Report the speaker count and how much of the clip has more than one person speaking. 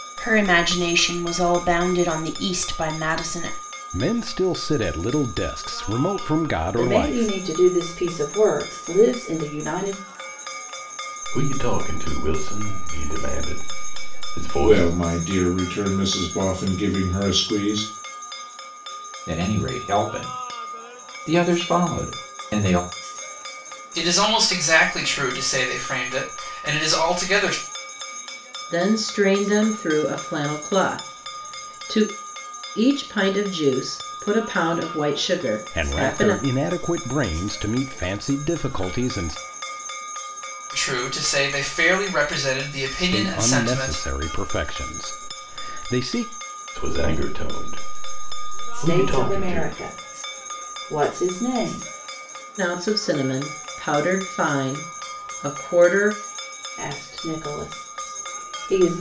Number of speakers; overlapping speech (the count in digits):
8, about 6%